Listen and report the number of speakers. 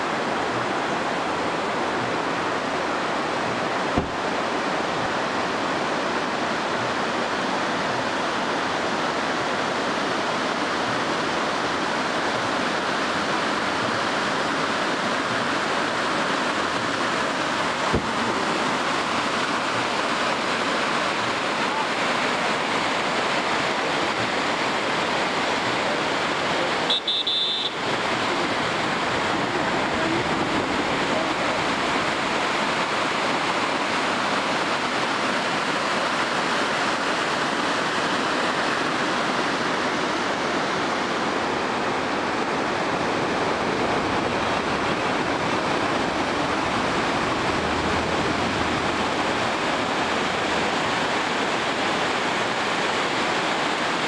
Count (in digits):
0